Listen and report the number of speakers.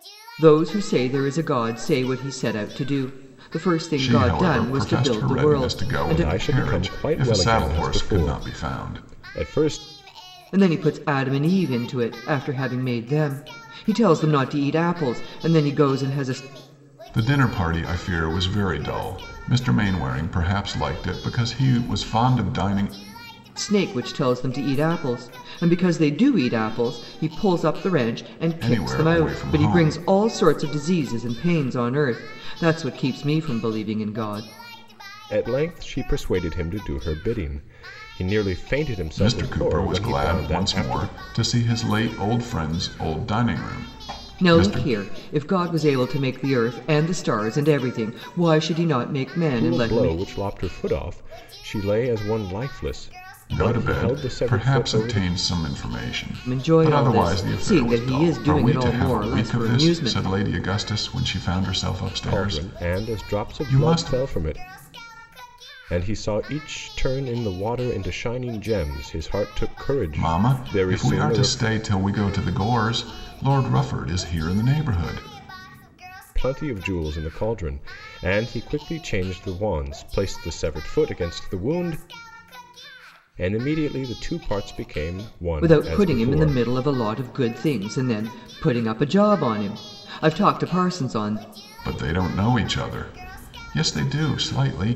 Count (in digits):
3